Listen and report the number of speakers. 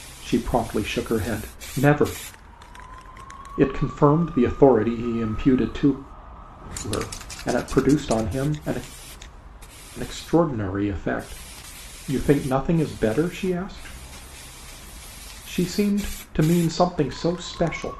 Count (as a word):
one